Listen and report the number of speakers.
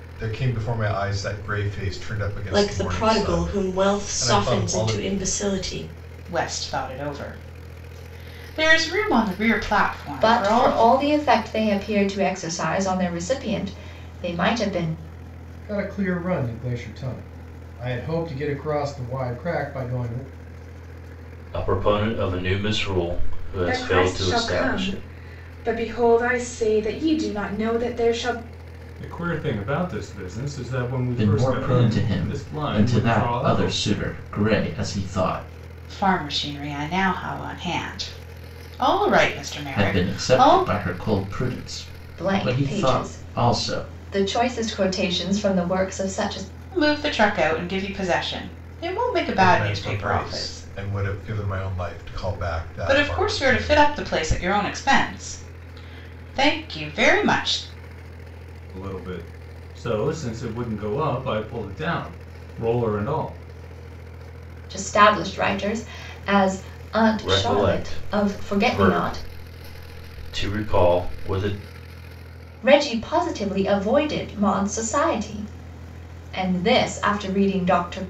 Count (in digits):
9